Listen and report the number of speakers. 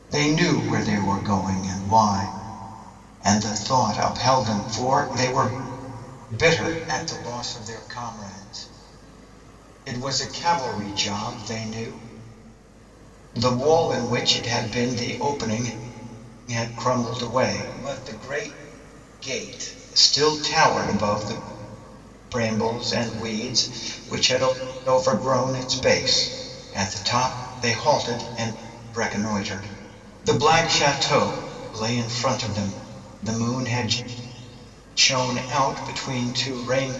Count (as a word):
one